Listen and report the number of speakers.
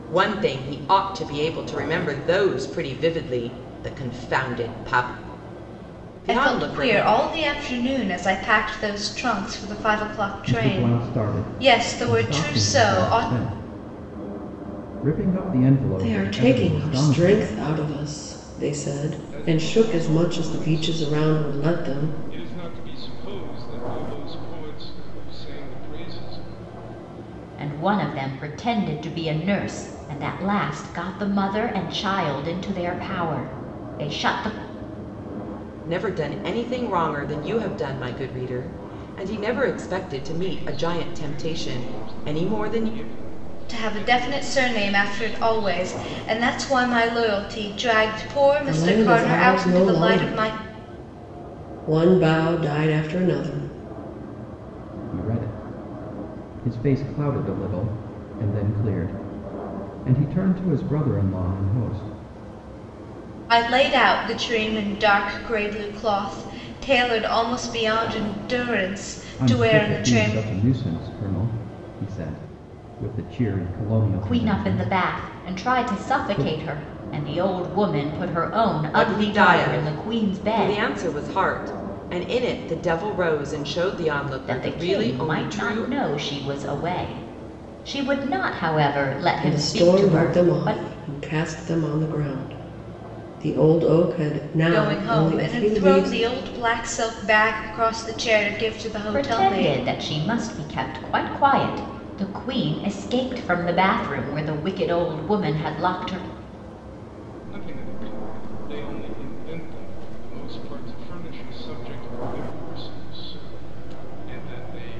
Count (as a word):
six